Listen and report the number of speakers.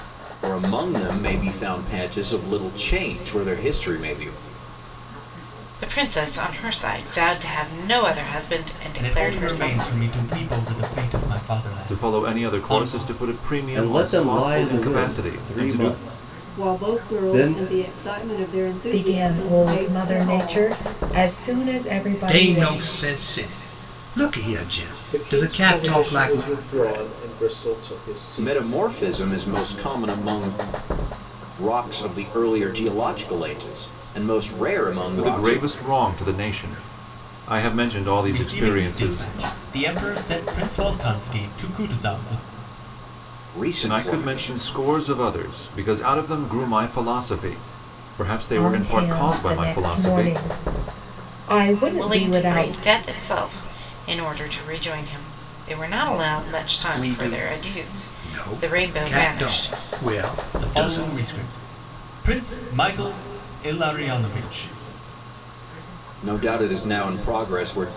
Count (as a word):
nine